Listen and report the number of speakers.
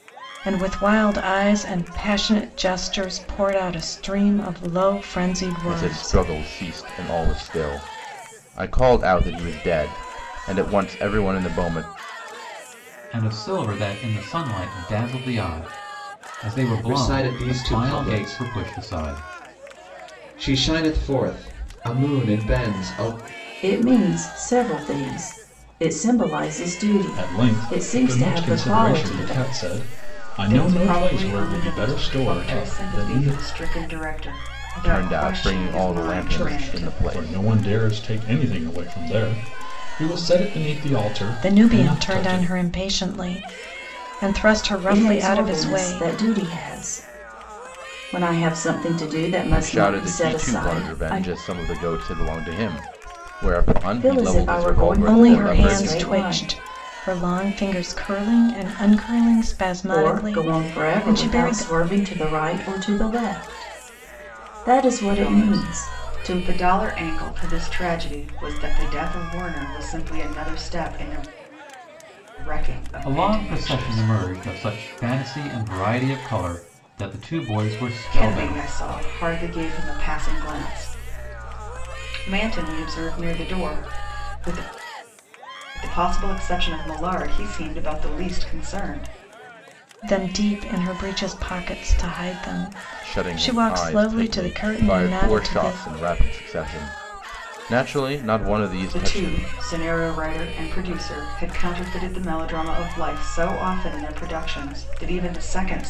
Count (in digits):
7